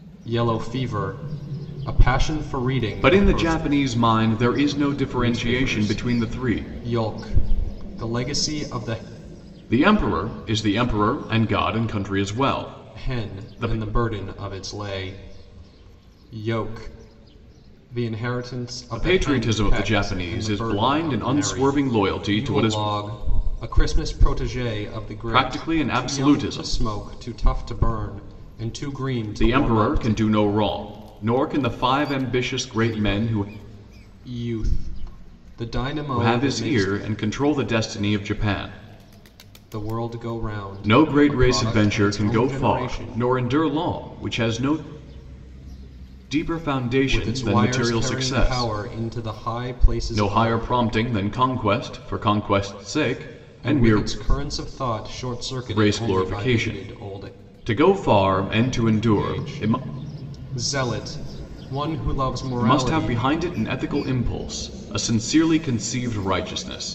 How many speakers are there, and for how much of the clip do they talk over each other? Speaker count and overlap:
two, about 28%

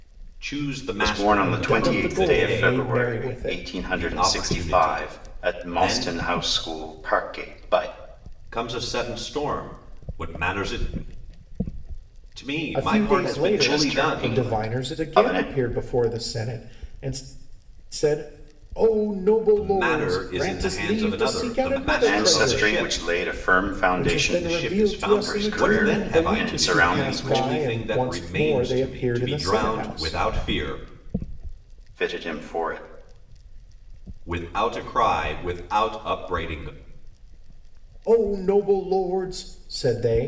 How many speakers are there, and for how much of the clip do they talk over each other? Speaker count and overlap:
three, about 43%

